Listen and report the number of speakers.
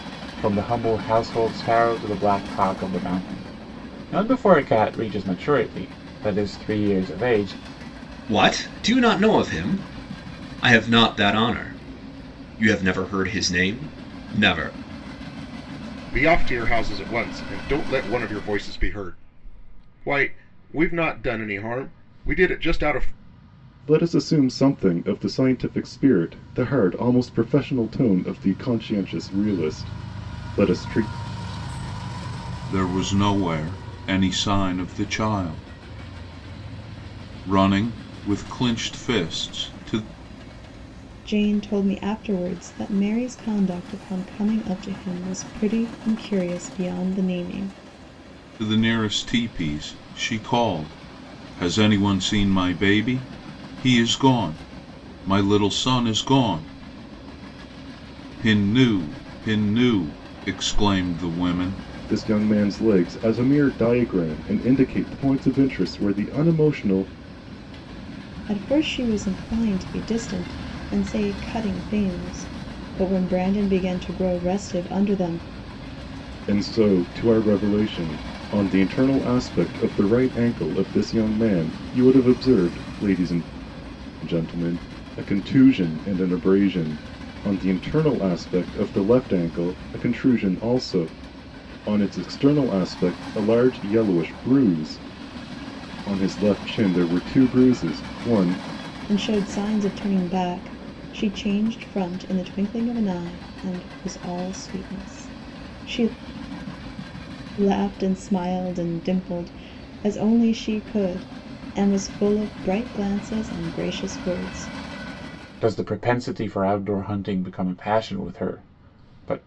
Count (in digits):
6